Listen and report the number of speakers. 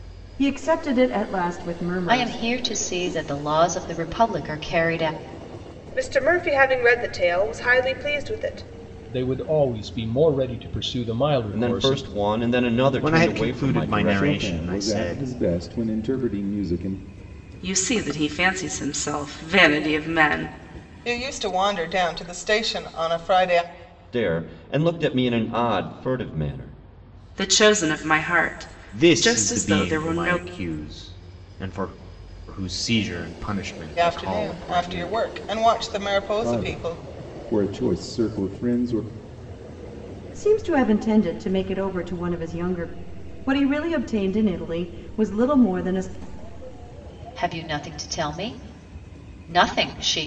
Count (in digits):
9